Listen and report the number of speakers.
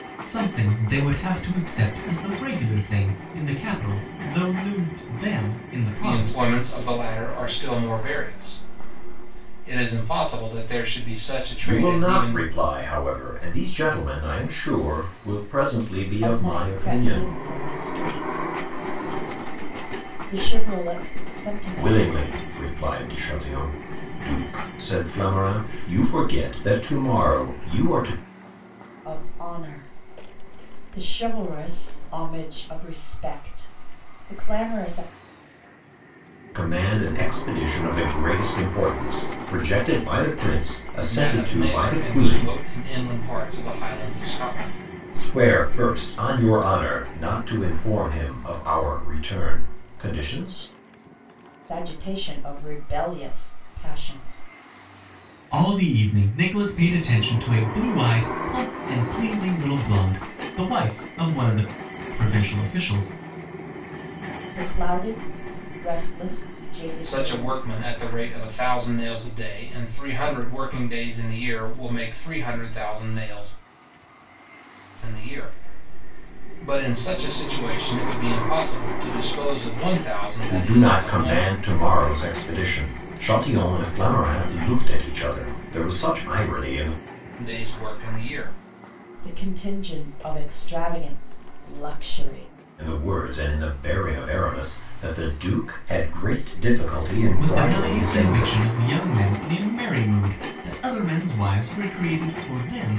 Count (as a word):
four